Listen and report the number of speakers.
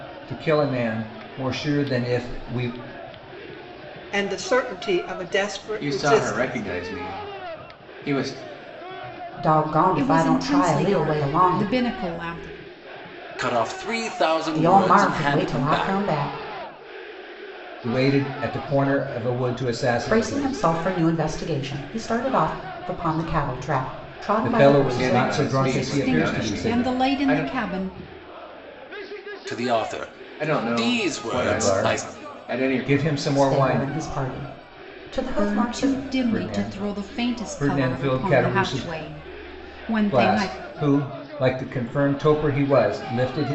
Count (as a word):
six